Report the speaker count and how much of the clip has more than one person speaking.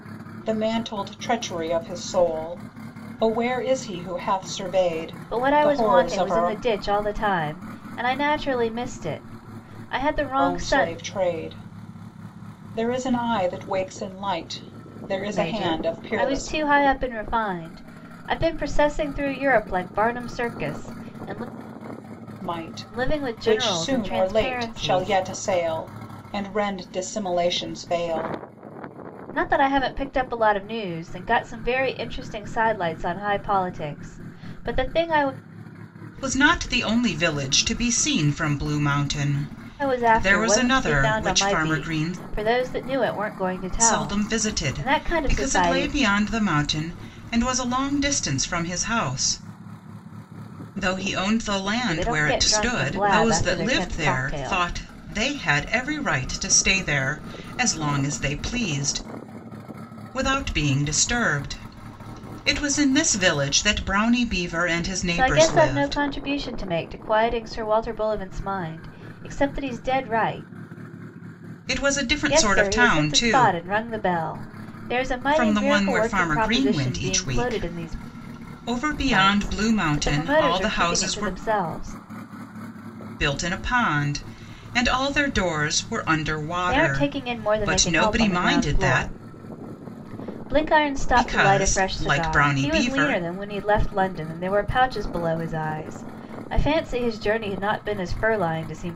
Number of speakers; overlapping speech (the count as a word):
two, about 25%